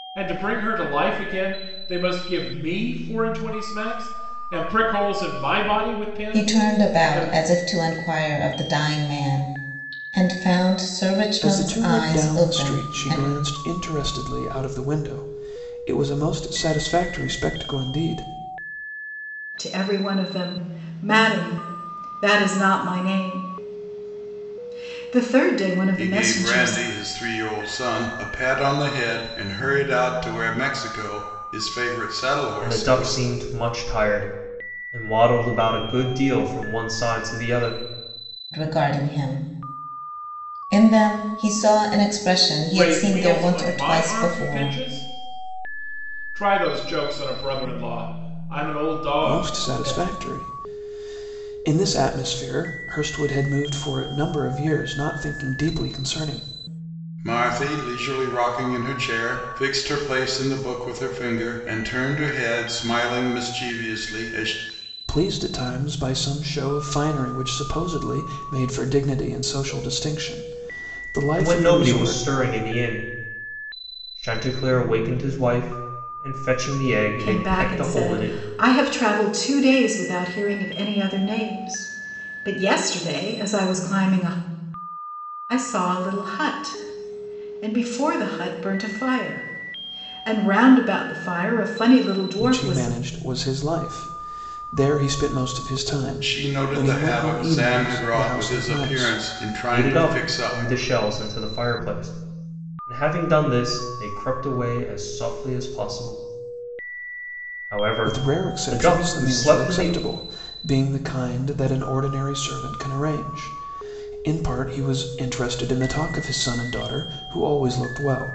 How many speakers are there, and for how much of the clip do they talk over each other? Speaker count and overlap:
6, about 14%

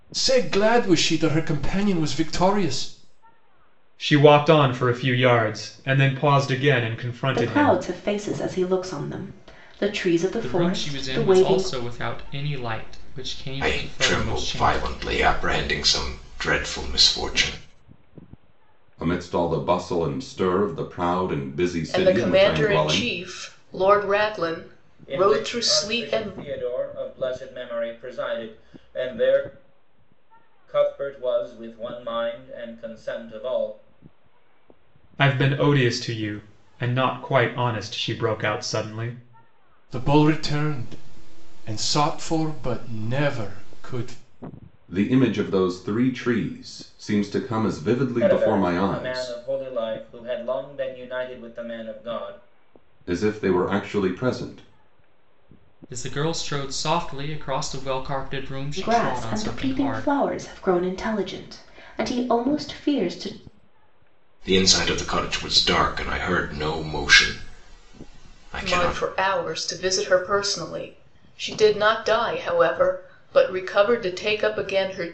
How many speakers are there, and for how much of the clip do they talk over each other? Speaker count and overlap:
8, about 12%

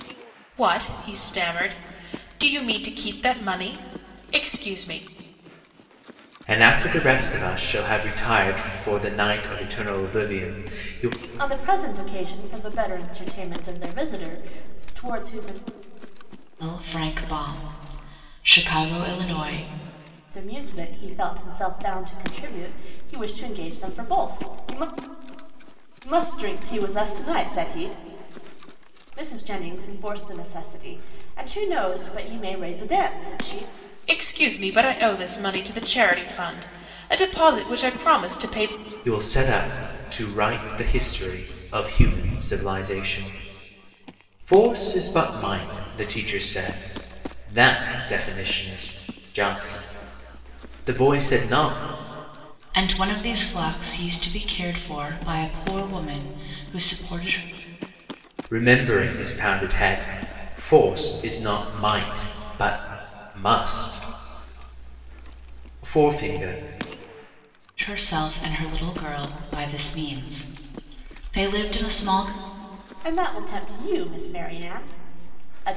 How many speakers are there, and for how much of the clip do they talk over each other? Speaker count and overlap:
4, no overlap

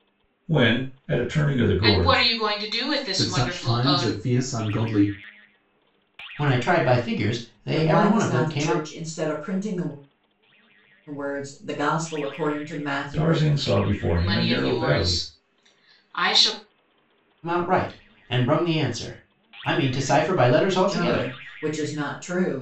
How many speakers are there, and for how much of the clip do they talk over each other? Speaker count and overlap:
5, about 20%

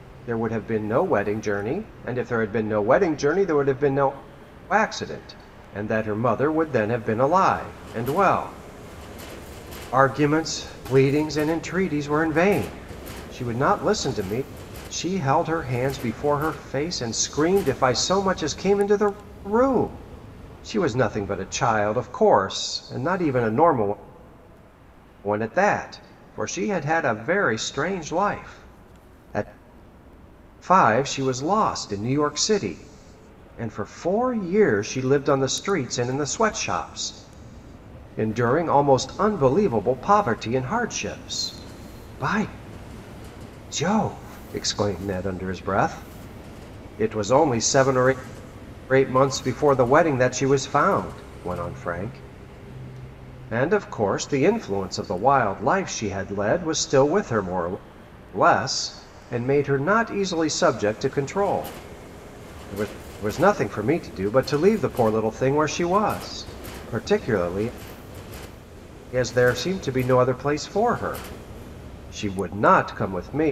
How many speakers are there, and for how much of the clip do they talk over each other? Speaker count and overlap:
1, no overlap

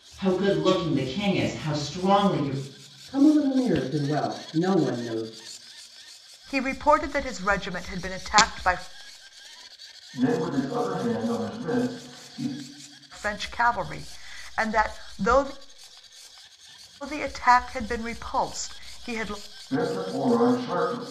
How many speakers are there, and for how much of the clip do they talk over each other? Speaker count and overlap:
4, no overlap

